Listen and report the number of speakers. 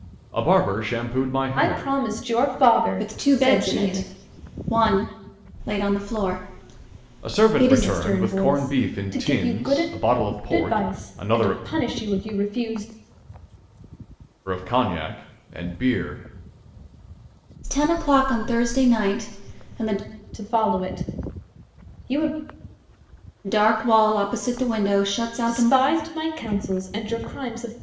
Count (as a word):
three